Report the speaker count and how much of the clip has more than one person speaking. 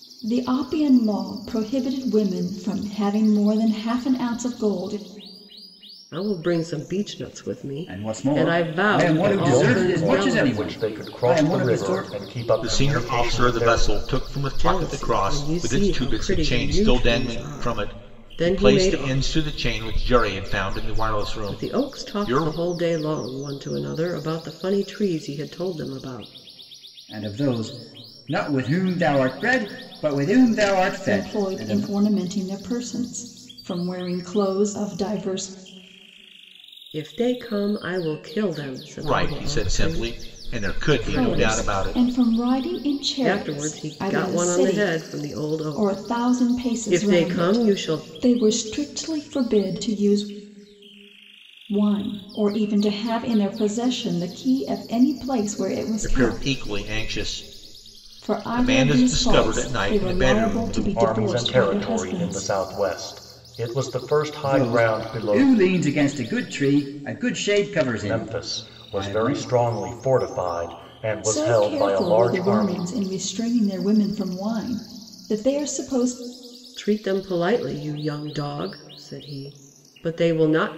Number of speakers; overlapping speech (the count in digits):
5, about 35%